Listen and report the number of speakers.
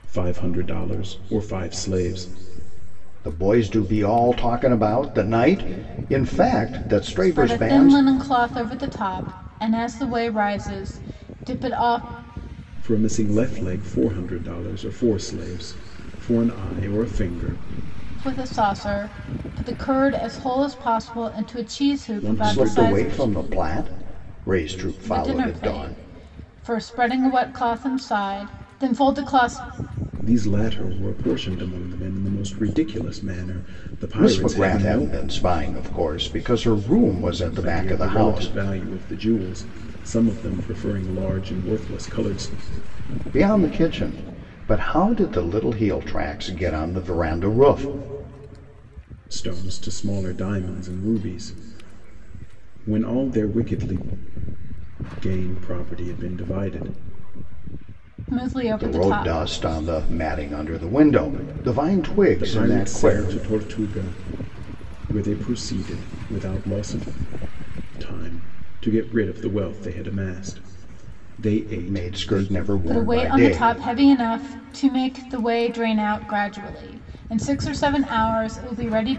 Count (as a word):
three